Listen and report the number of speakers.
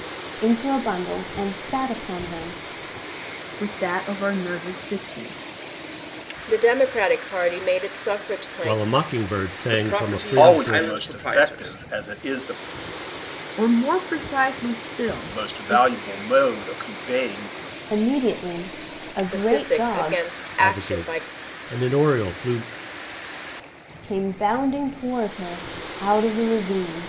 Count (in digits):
6